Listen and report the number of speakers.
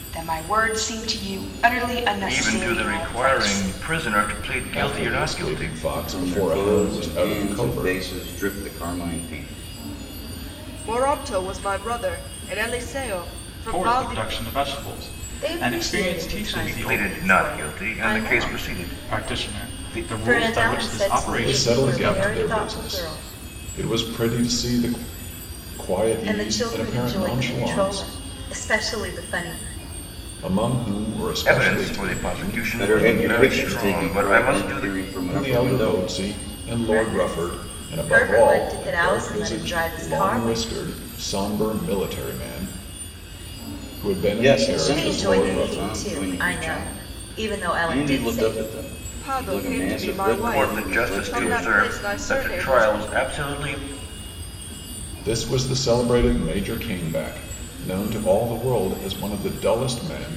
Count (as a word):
seven